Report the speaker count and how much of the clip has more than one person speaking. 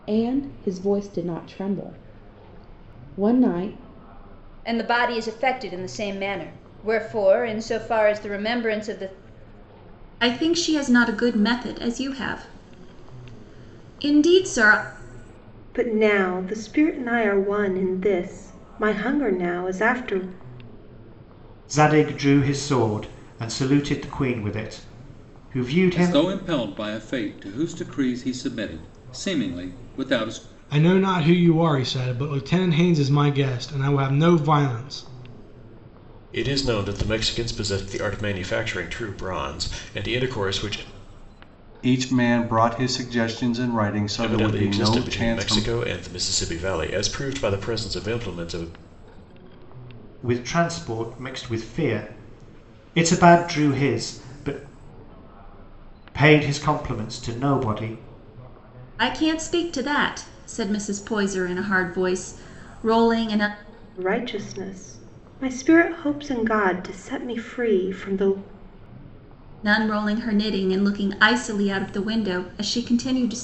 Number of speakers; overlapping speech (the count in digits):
9, about 2%